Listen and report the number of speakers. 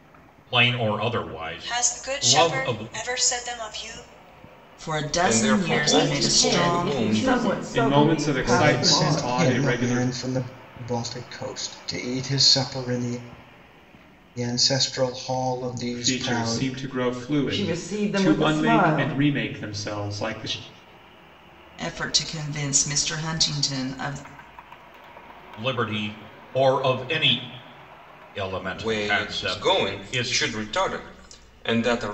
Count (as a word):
eight